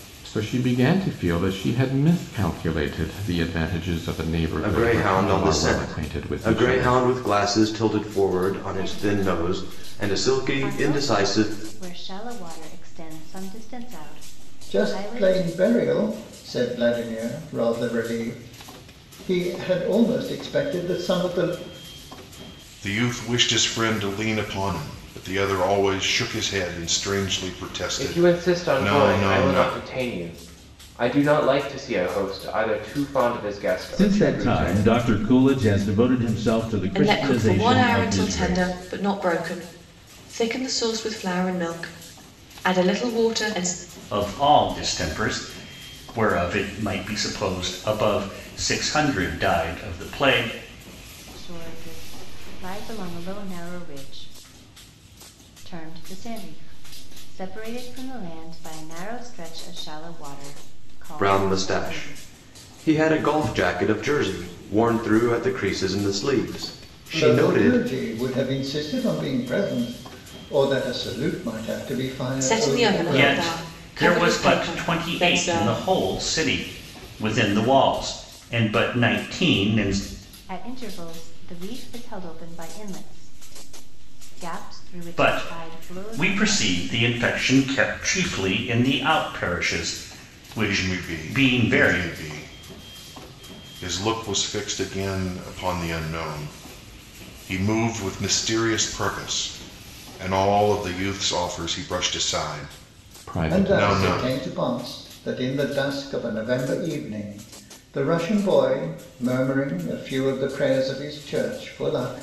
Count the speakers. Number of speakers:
nine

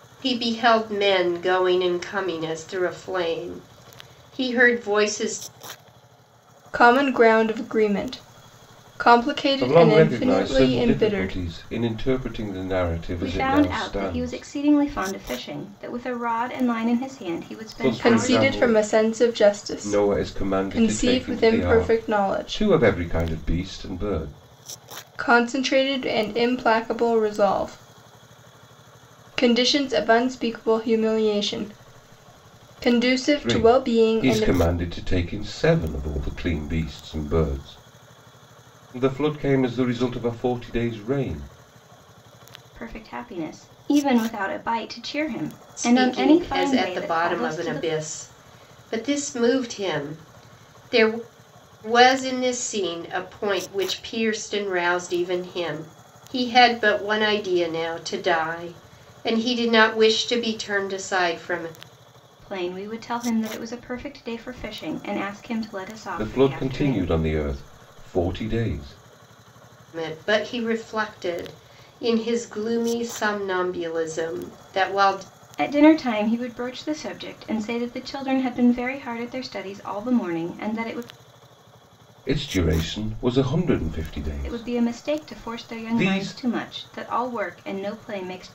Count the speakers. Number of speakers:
four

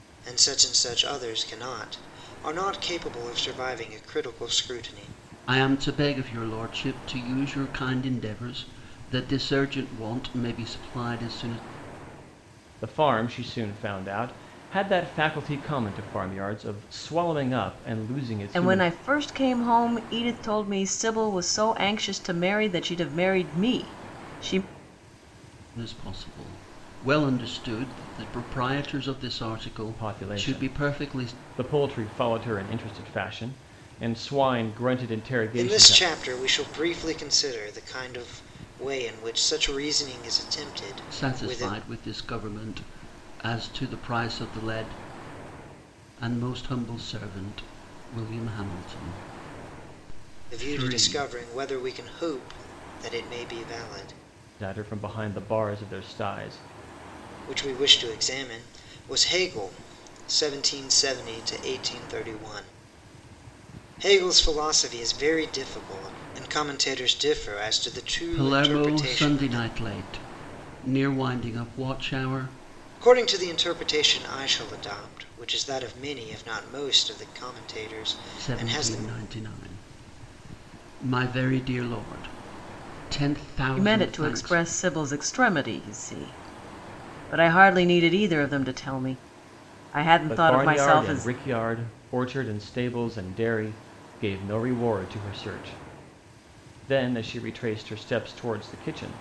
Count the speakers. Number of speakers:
four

